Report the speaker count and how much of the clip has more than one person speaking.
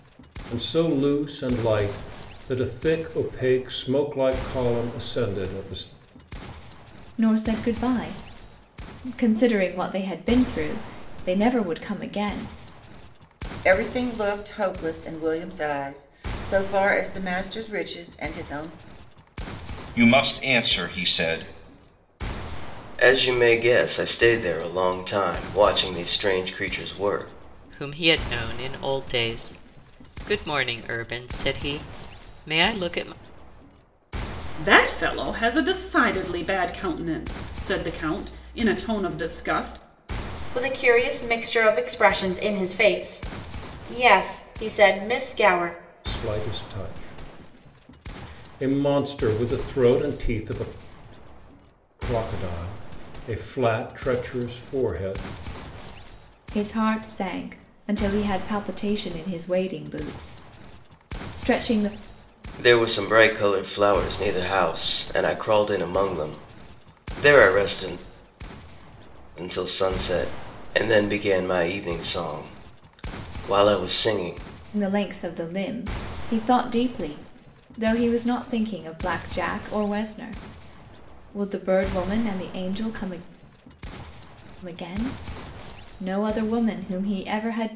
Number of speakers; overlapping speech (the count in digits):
8, no overlap